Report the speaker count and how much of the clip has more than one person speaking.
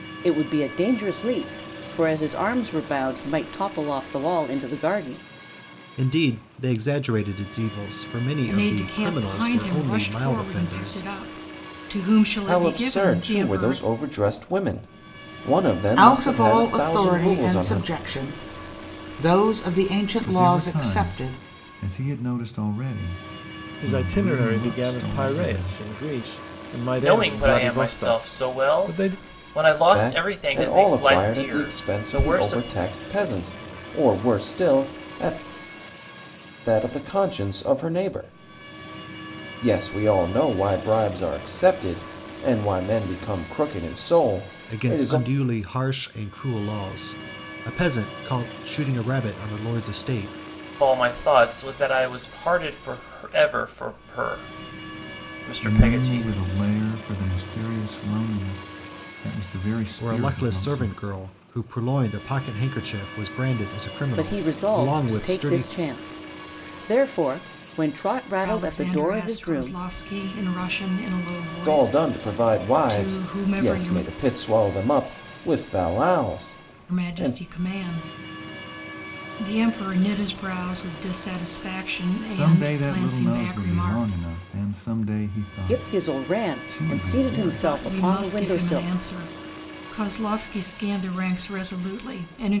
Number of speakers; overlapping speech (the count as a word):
eight, about 30%